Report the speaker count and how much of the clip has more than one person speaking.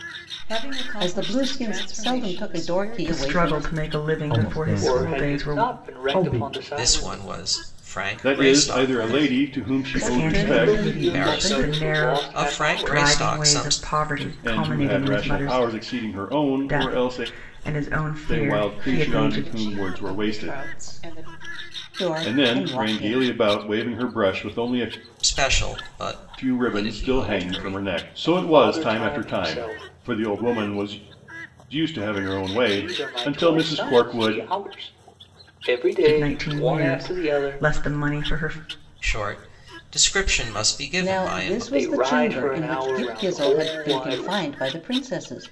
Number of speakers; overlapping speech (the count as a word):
seven, about 59%